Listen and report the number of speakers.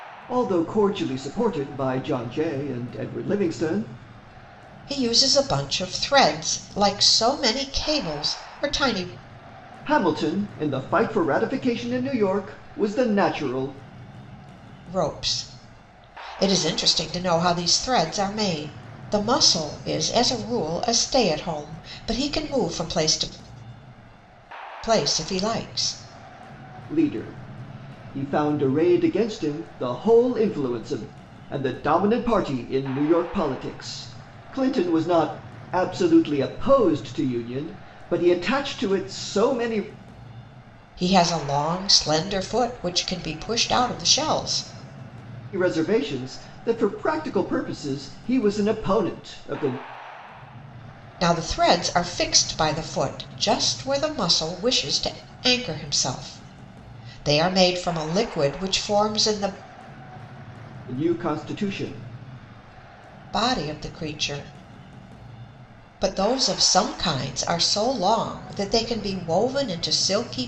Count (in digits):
2